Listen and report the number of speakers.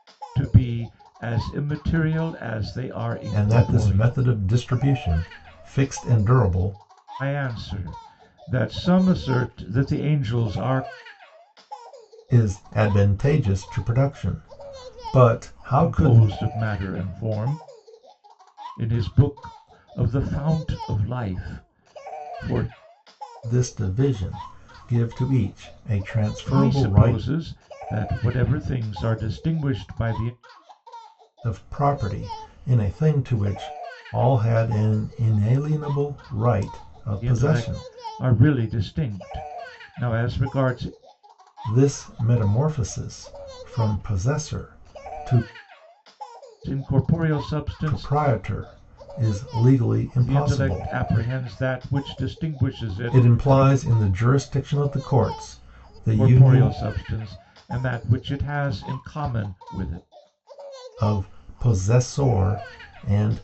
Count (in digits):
2